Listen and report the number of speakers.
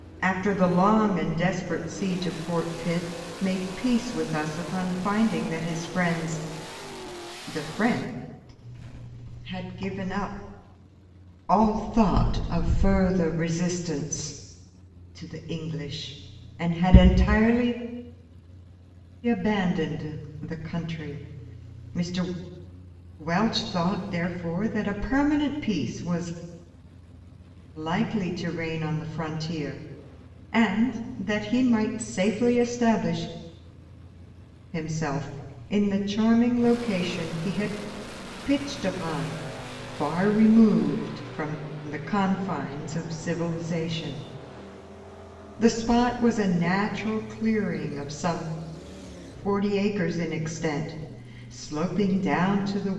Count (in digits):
1